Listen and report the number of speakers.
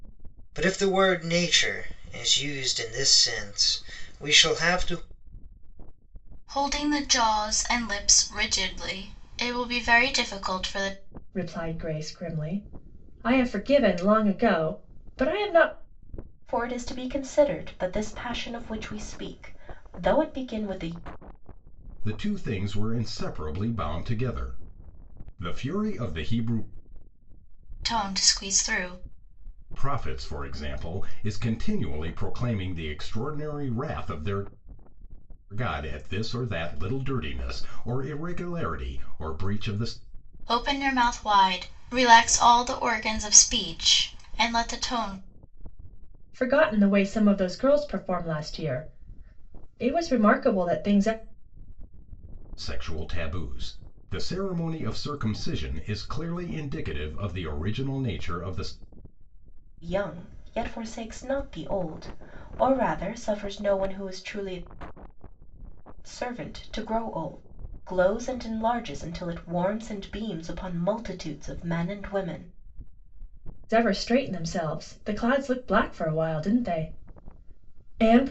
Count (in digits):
5